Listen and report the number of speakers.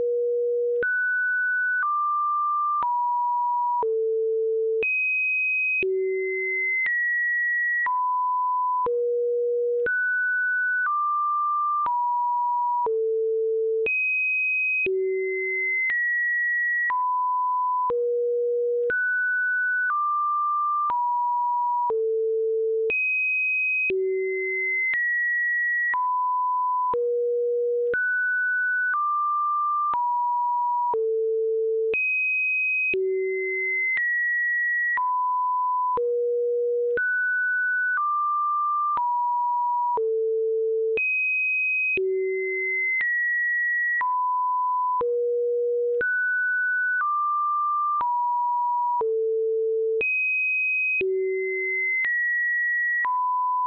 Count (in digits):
0